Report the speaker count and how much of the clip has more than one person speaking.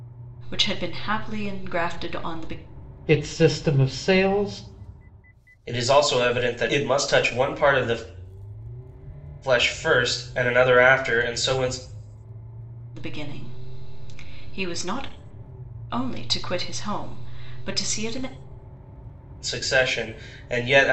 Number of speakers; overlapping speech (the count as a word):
three, no overlap